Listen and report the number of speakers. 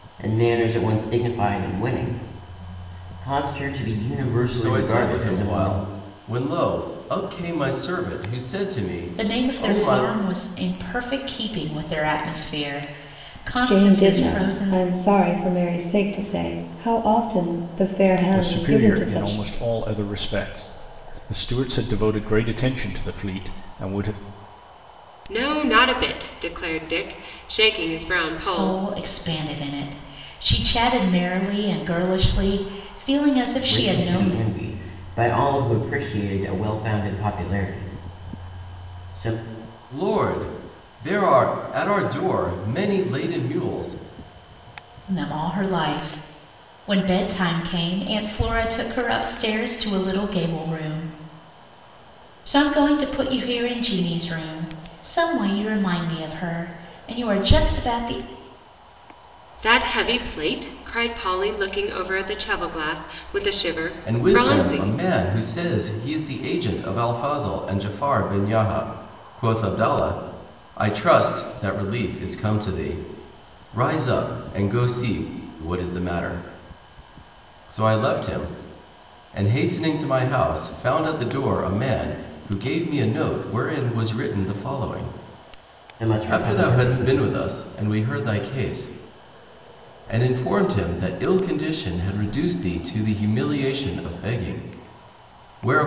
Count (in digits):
6